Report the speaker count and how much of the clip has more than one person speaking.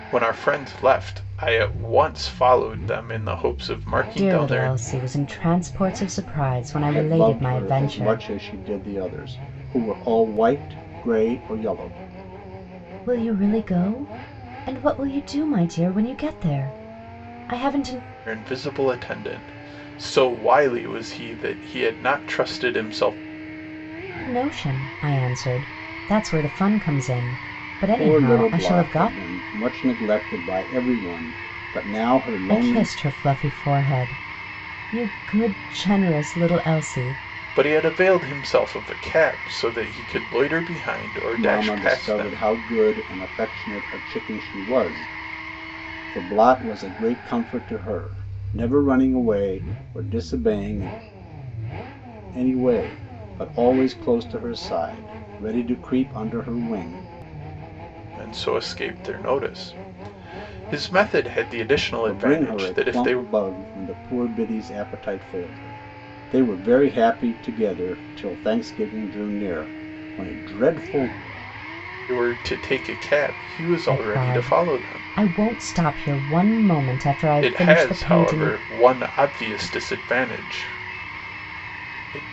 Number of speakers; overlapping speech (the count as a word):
three, about 10%